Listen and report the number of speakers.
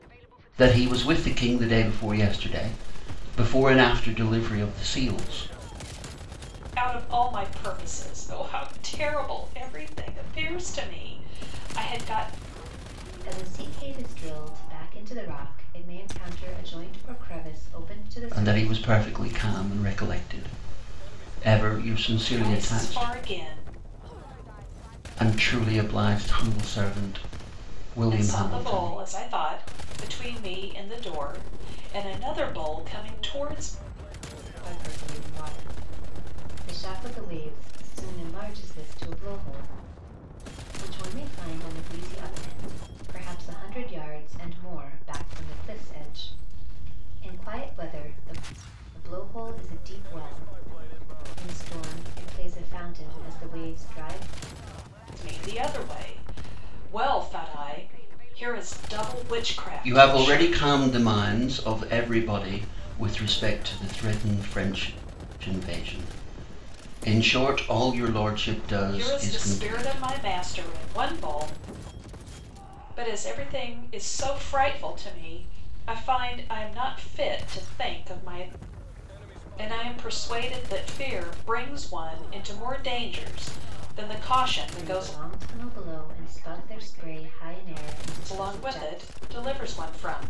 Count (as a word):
three